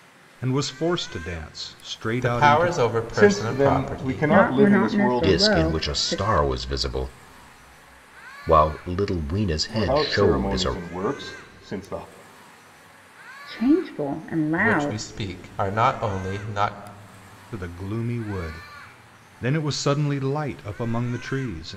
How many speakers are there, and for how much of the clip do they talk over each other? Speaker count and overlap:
5, about 25%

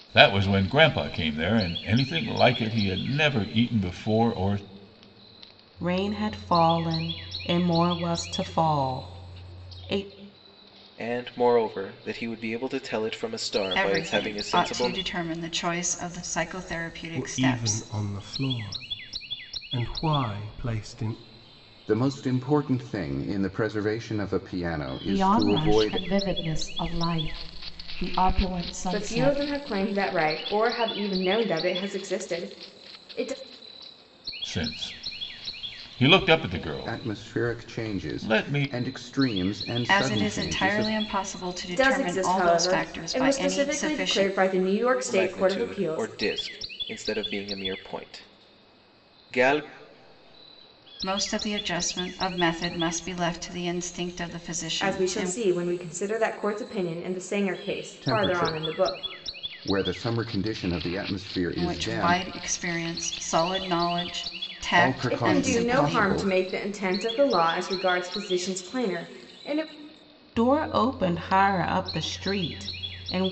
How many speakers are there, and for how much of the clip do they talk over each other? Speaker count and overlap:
8, about 20%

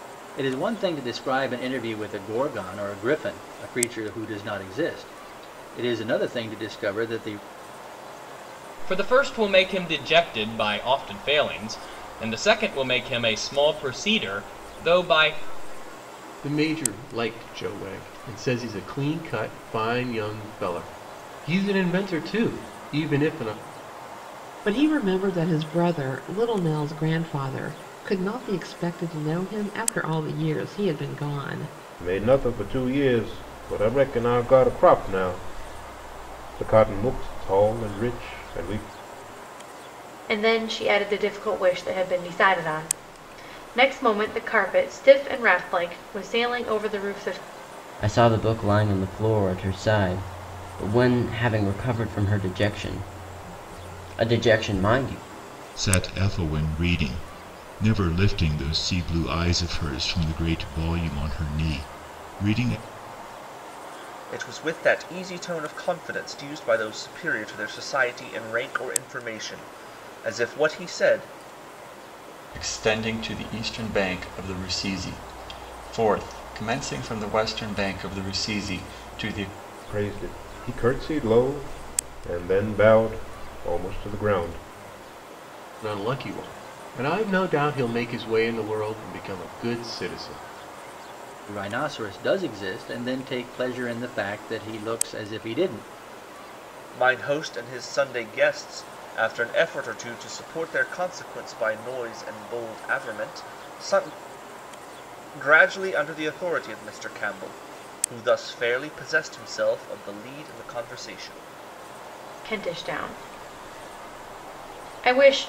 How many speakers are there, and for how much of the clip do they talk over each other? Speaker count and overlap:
10, no overlap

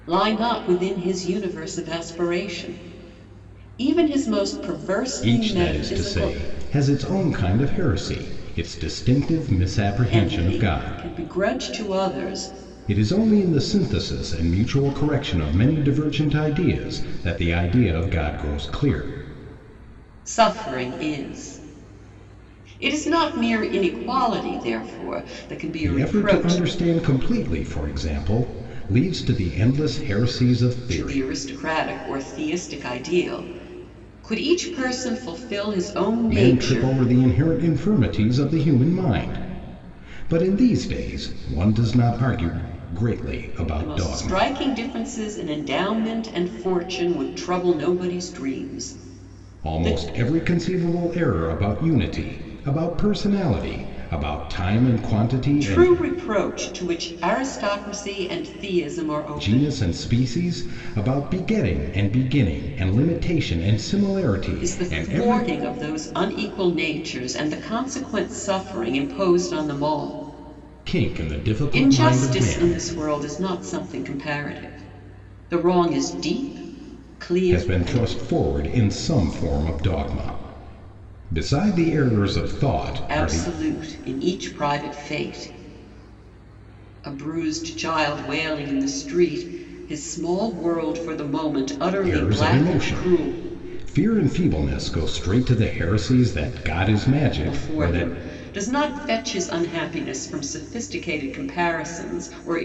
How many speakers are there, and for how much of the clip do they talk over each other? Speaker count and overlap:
2, about 11%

